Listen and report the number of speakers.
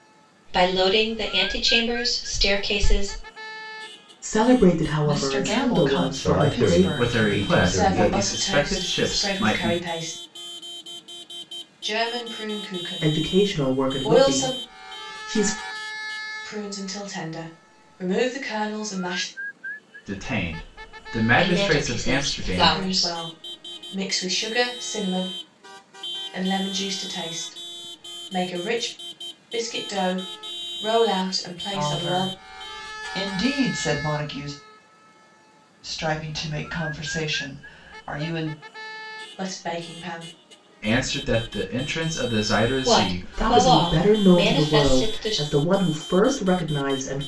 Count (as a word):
six